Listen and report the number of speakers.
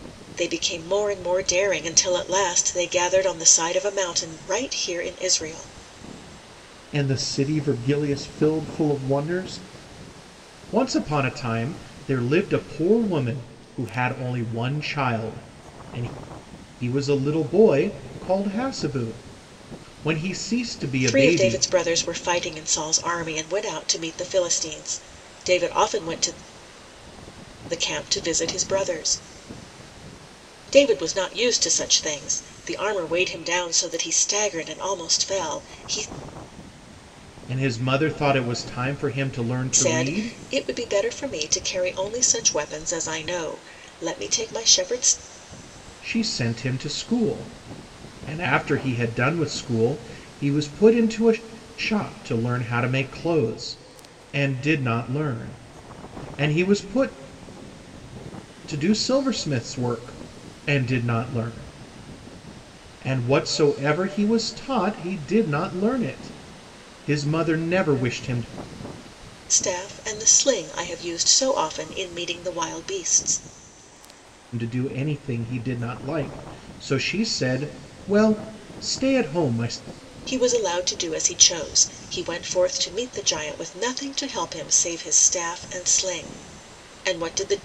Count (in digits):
2